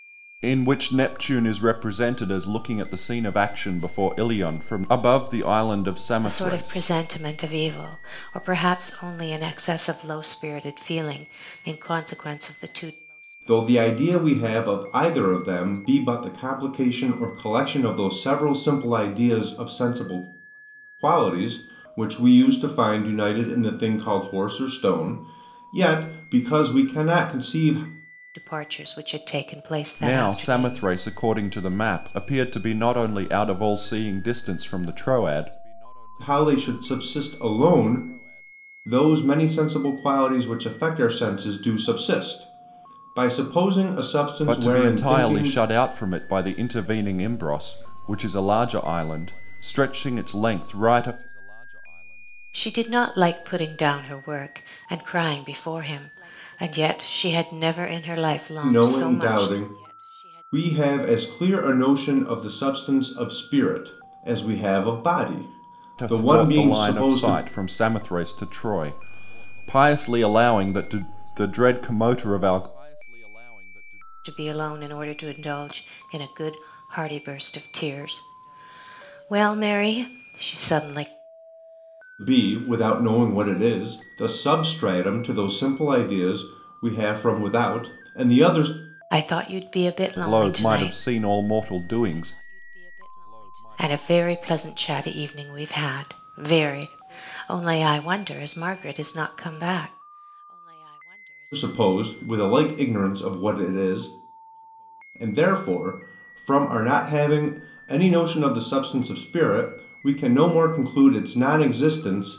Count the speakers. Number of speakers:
3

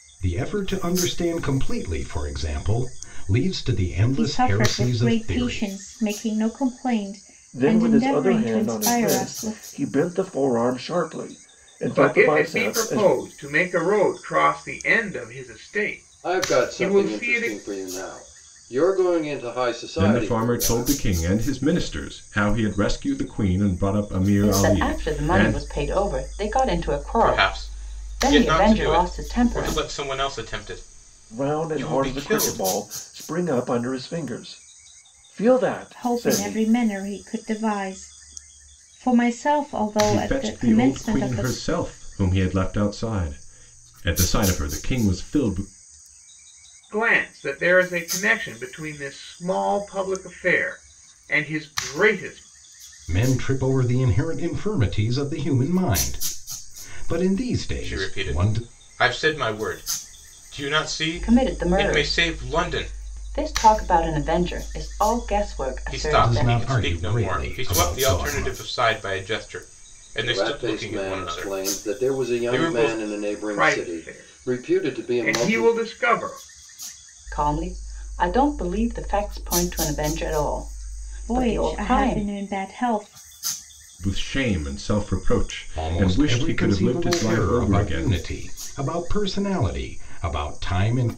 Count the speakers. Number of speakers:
8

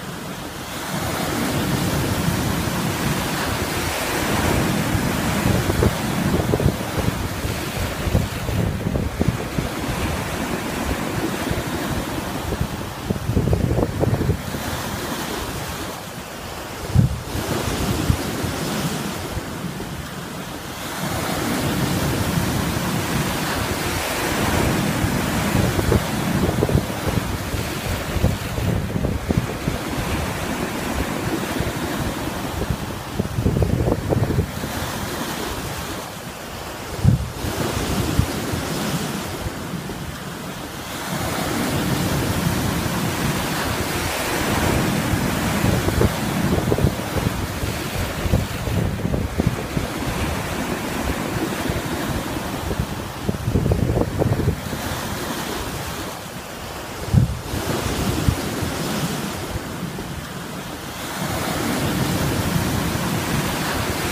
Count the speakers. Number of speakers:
0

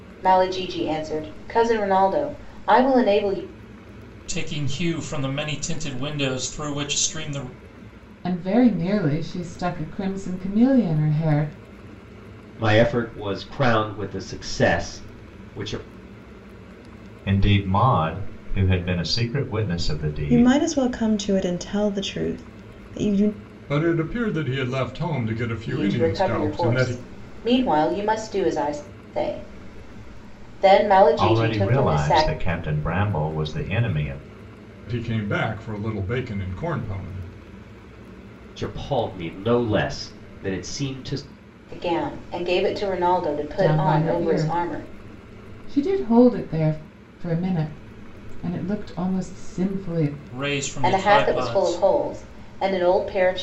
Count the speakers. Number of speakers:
7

